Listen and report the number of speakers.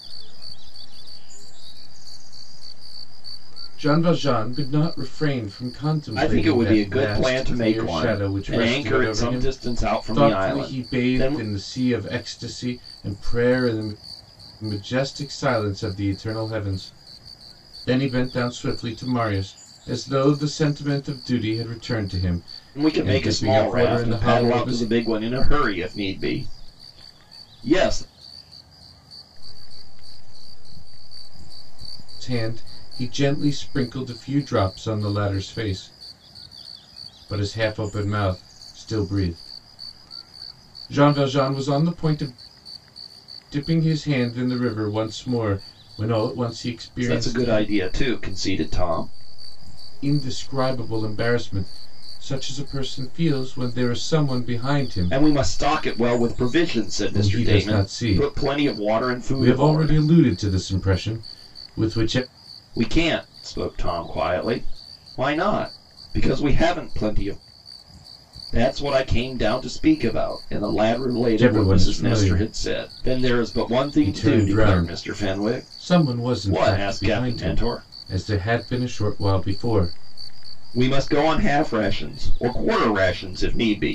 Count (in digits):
3